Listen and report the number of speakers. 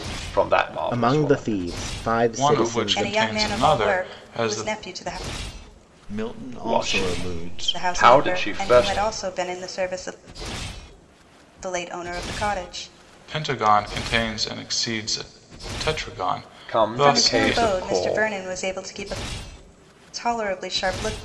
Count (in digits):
5